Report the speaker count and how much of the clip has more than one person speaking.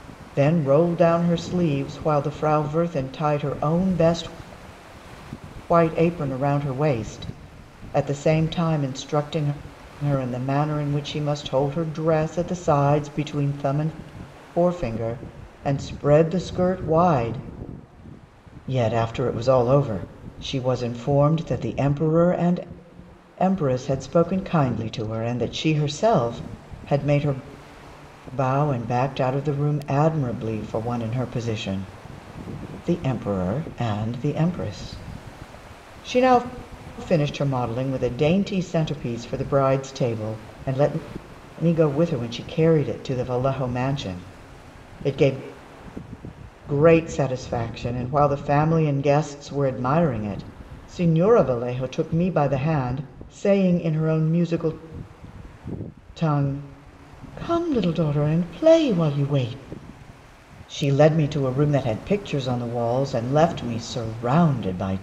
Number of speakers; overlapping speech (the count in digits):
1, no overlap